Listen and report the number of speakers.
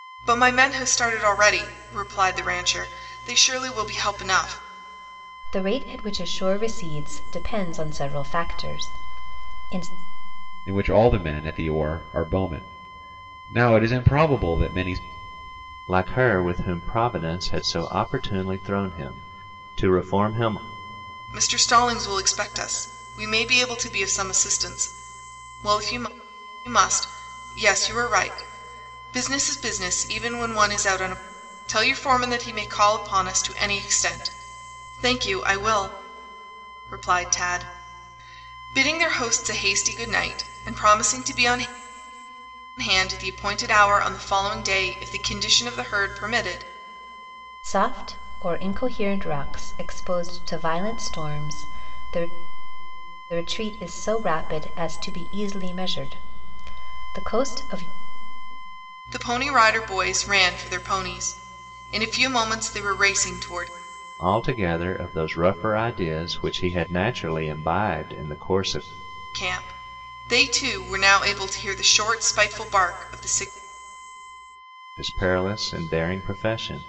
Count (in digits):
4